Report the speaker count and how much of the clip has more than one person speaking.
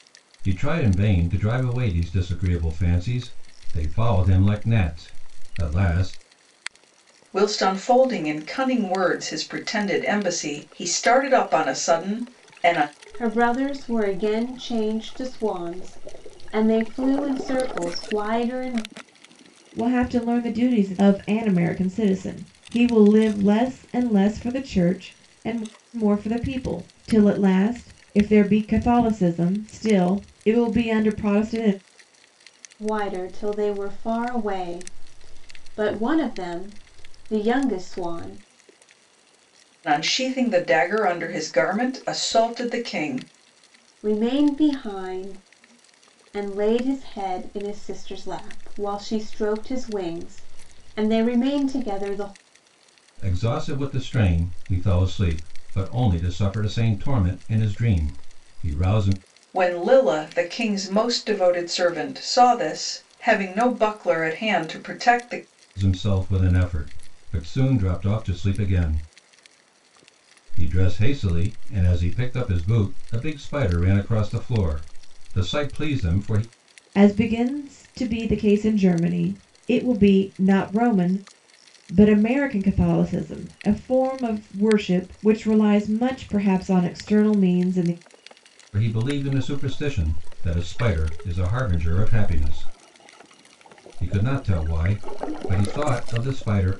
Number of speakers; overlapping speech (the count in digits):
4, no overlap